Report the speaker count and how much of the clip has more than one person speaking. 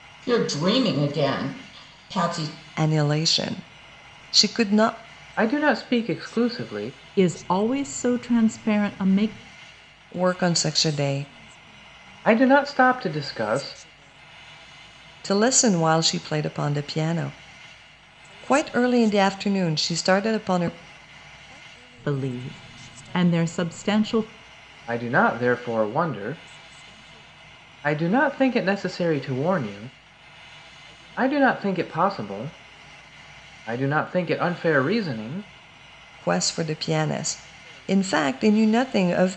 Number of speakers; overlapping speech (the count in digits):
4, no overlap